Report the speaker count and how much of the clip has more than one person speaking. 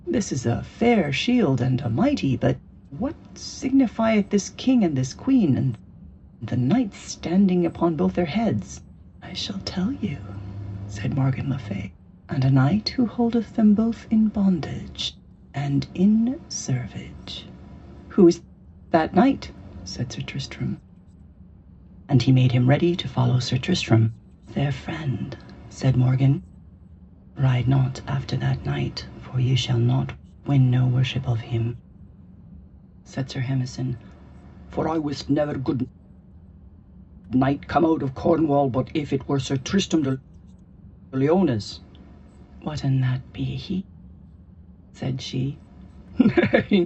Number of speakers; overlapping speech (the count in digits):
1, no overlap